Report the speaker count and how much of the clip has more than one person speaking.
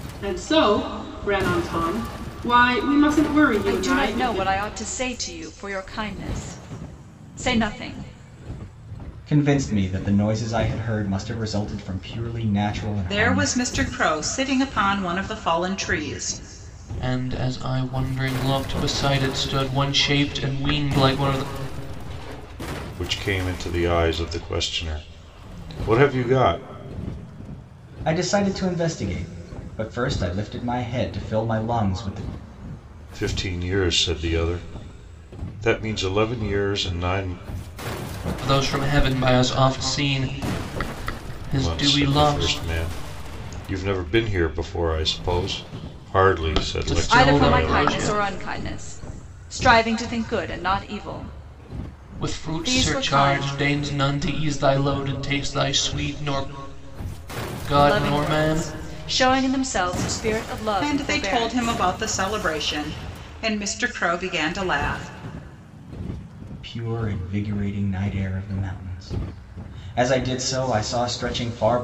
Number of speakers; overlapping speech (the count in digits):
6, about 10%